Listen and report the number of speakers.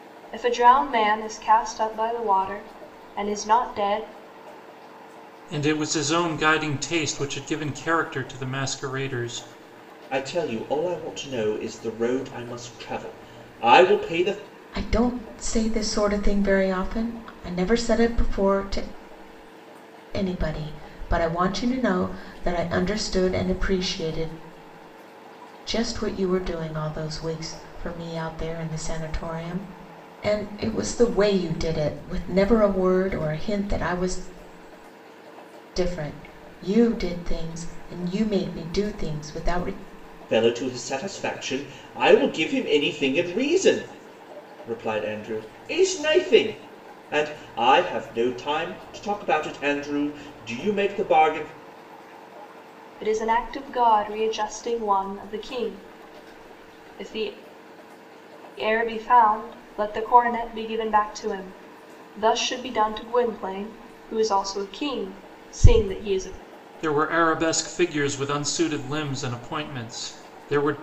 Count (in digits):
4